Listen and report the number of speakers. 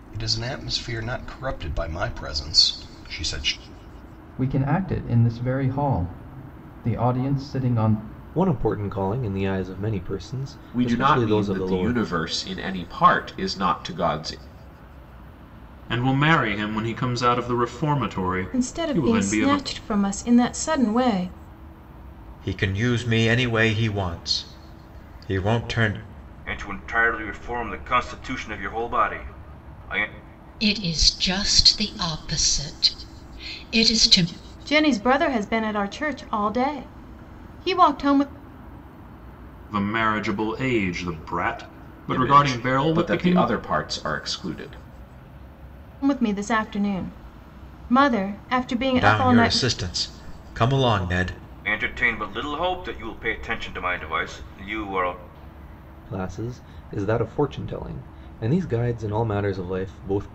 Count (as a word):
nine